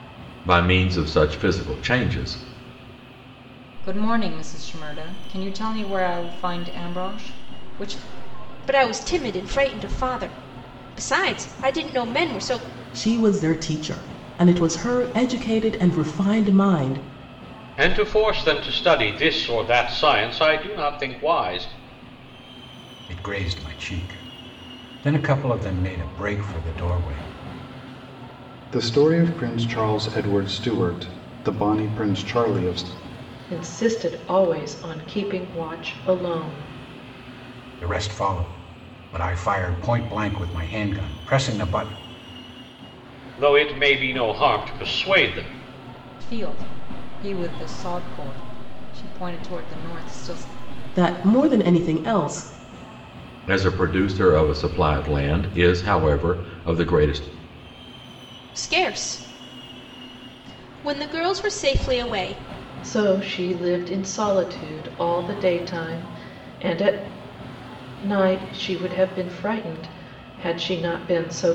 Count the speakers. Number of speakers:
8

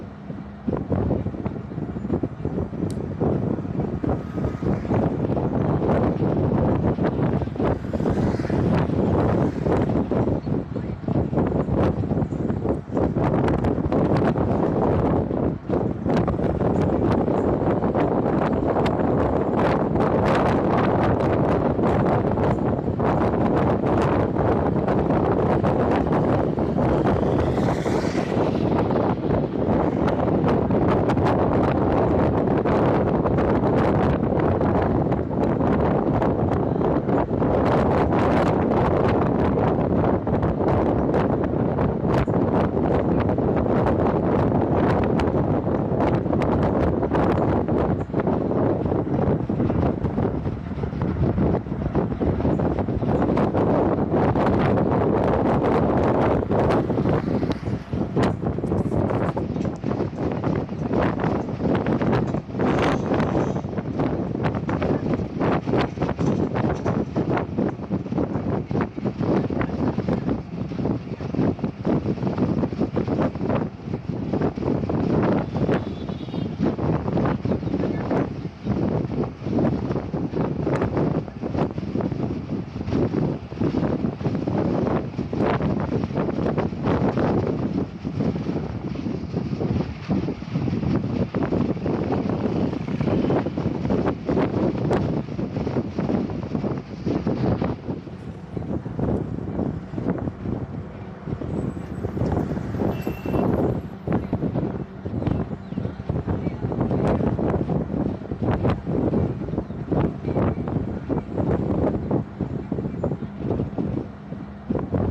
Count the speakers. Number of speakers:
0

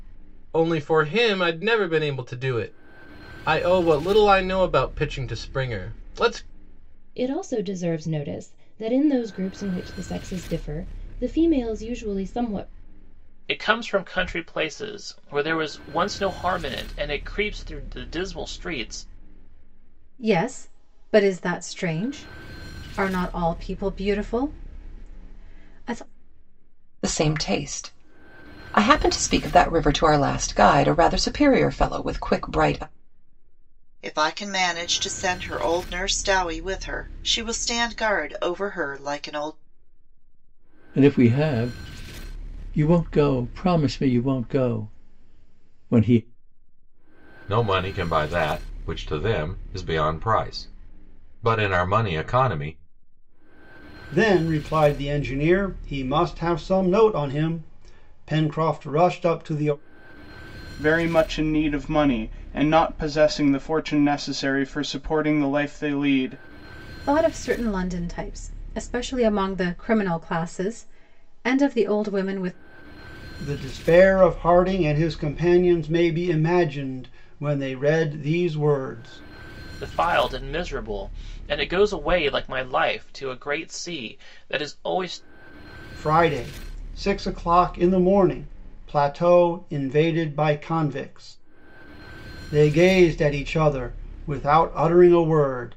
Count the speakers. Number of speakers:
10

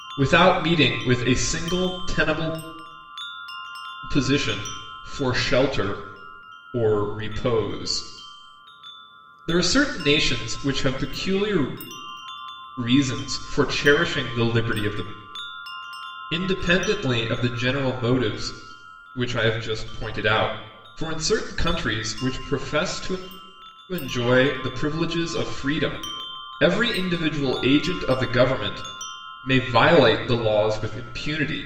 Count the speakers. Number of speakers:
1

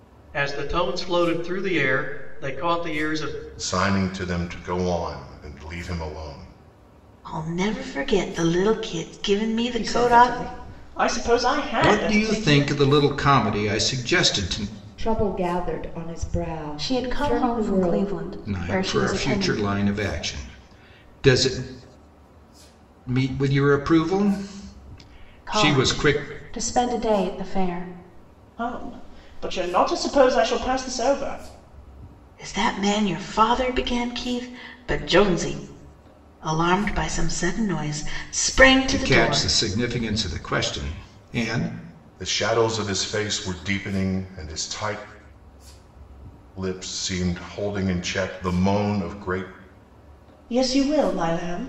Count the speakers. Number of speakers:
7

